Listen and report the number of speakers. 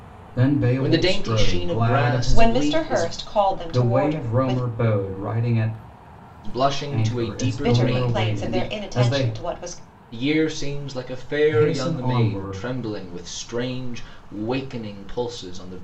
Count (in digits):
3